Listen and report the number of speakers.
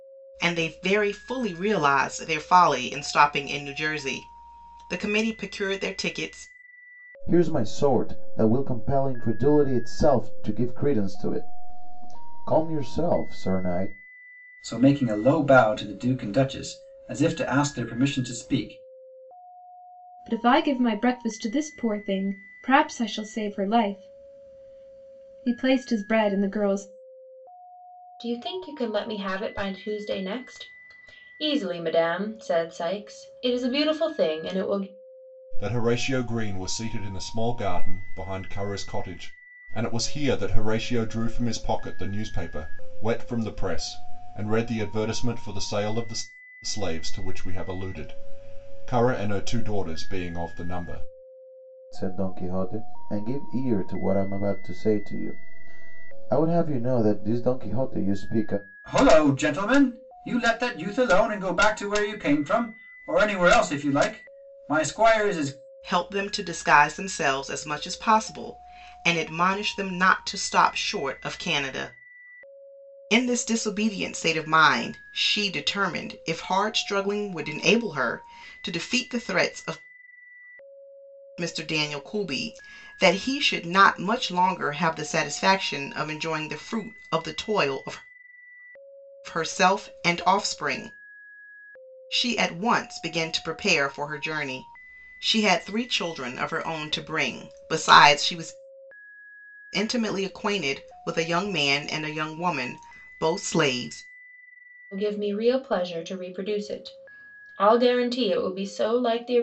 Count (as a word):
six